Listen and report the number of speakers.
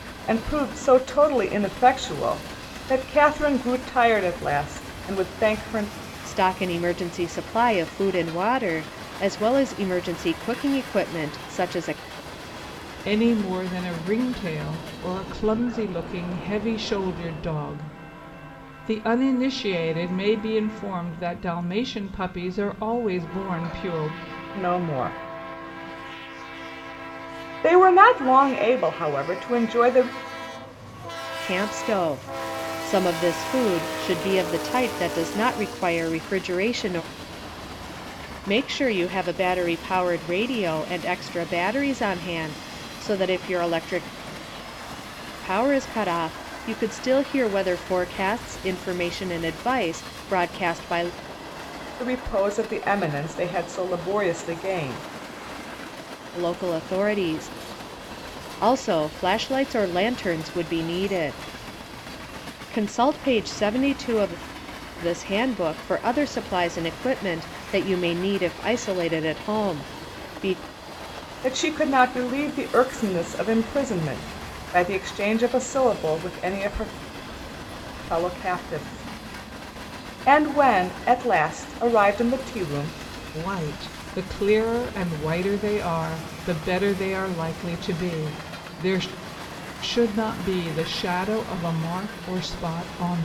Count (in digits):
3